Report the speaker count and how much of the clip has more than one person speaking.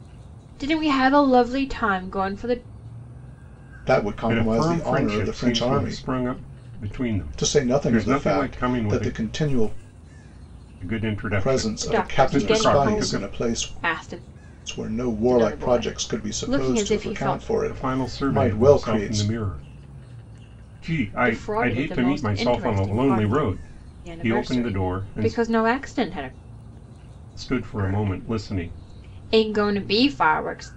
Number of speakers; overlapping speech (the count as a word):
three, about 47%